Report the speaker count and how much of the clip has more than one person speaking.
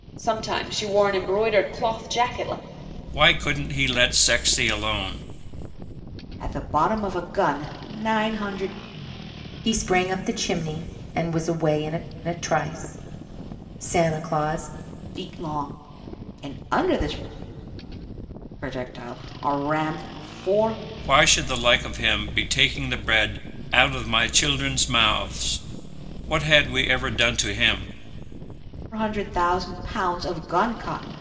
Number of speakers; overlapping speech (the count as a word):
four, no overlap